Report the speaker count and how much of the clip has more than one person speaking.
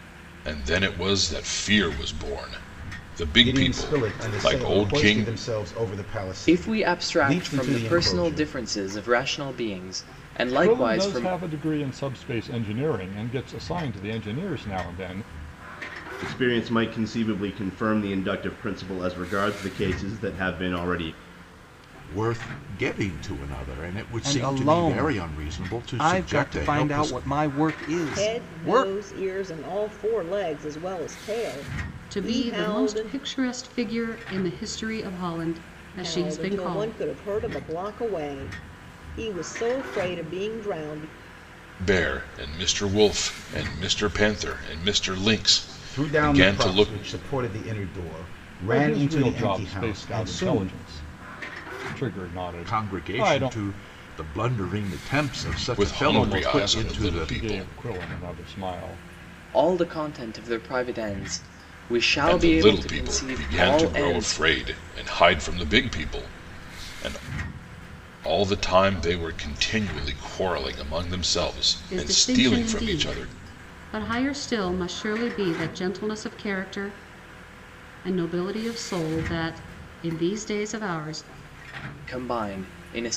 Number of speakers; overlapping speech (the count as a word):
nine, about 25%